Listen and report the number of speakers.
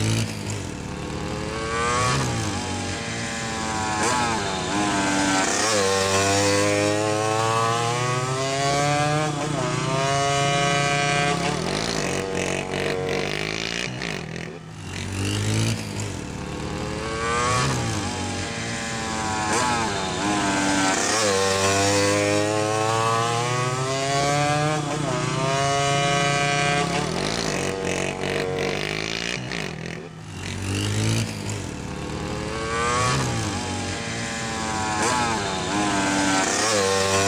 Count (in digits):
0